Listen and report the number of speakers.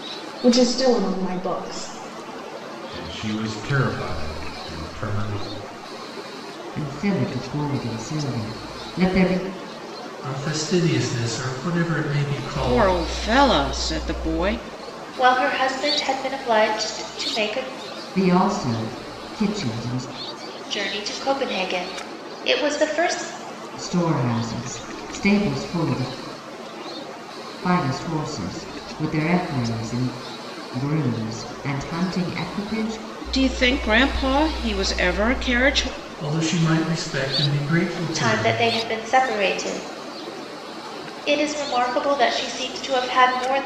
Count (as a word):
six